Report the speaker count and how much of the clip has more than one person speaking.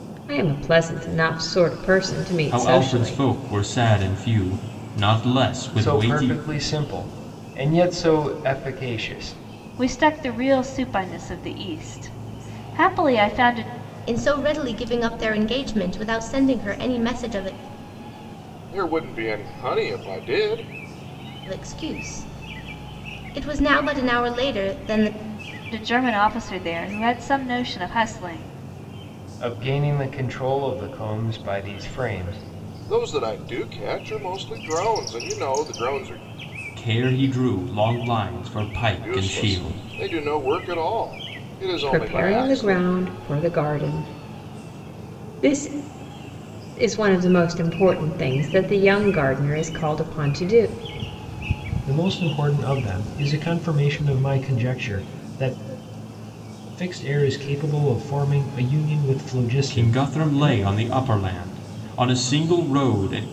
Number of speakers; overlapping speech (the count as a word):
six, about 7%